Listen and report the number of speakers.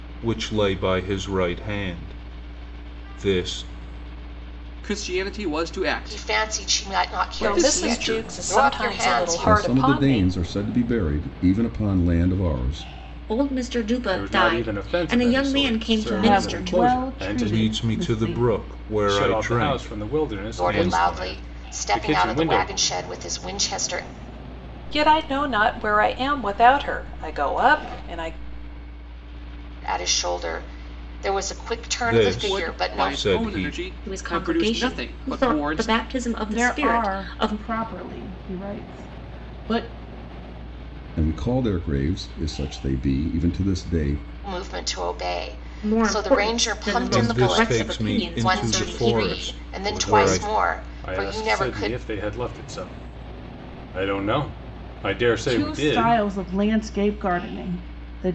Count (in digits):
8